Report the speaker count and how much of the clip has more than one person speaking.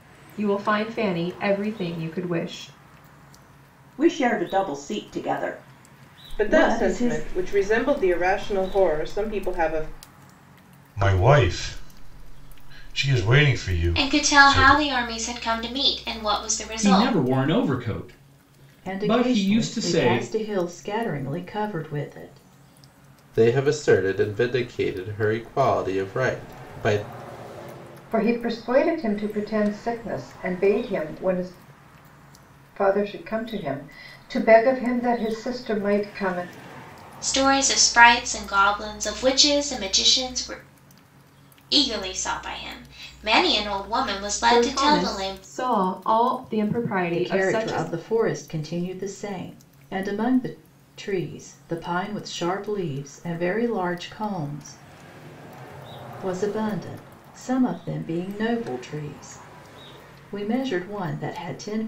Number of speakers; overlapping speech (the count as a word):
nine, about 9%